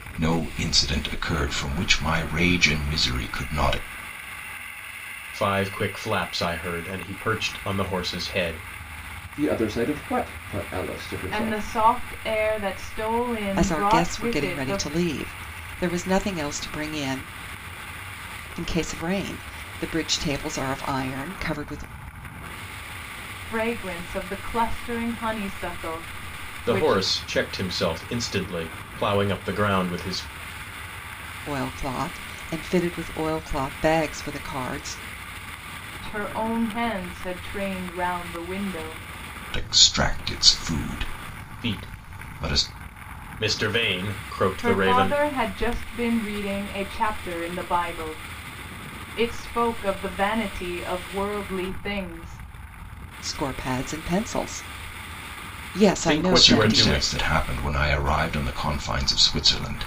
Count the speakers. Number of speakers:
5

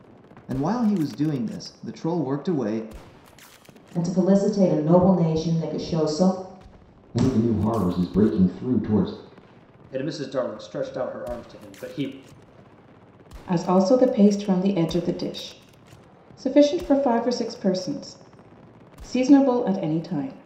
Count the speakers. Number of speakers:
5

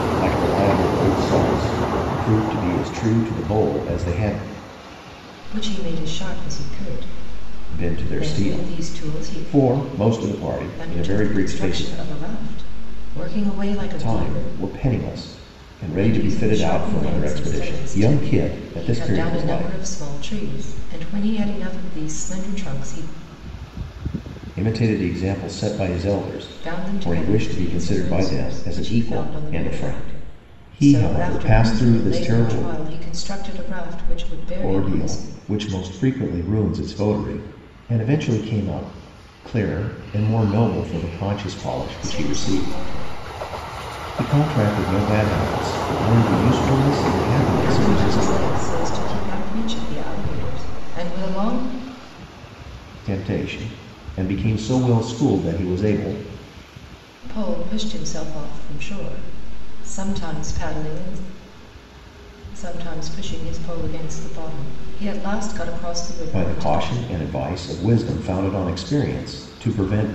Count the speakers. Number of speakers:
2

